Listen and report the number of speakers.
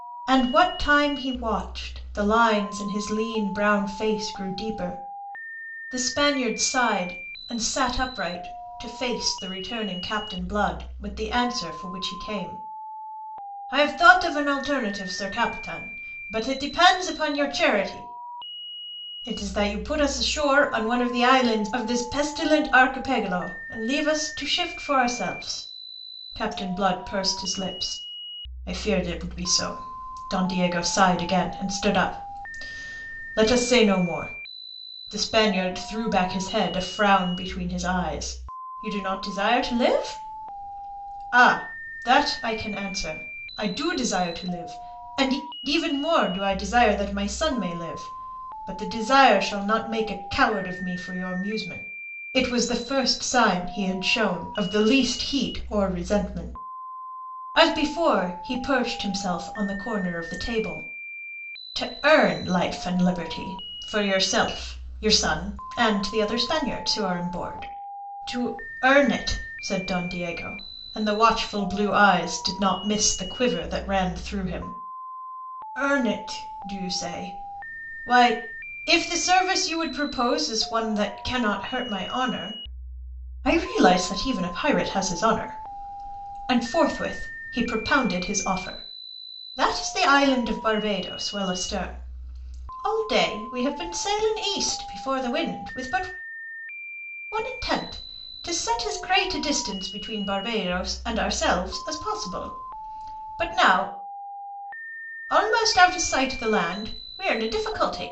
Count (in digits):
1